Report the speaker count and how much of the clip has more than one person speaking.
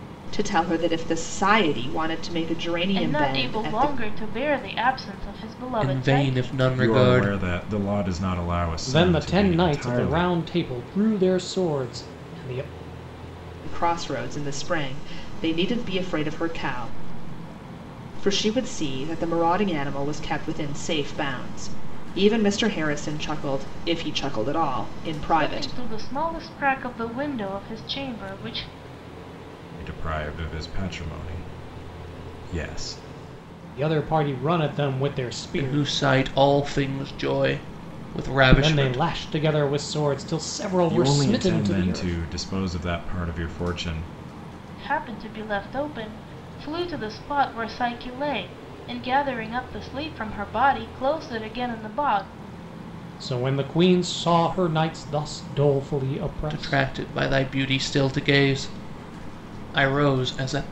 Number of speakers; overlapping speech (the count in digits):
5, about 12%